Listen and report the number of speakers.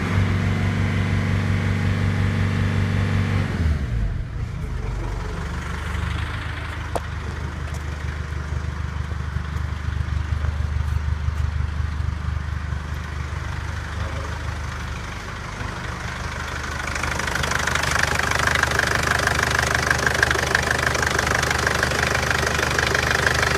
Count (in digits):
0